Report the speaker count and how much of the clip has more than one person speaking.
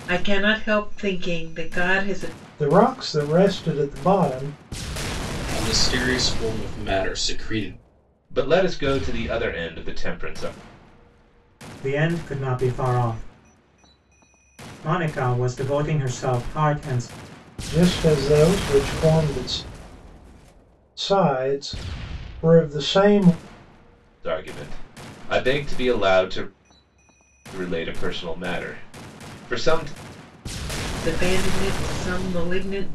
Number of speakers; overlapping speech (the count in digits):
5, no overlap